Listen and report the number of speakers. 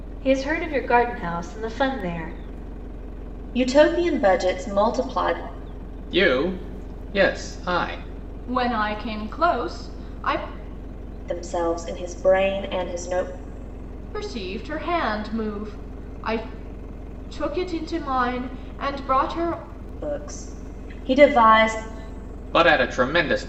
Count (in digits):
4